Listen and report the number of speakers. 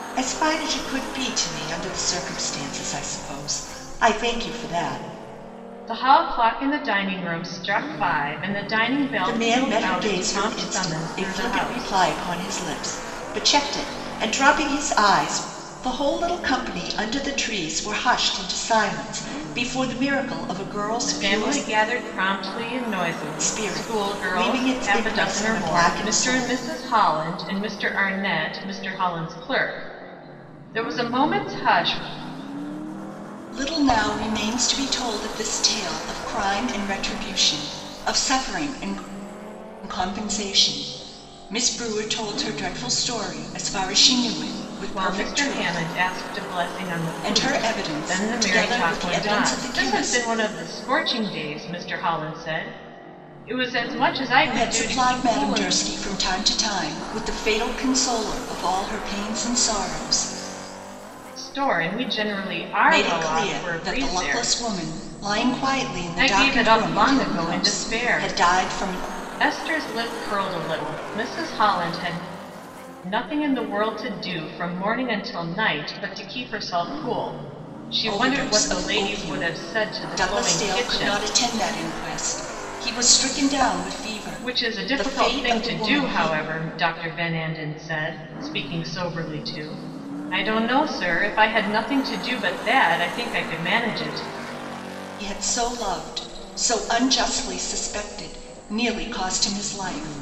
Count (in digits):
2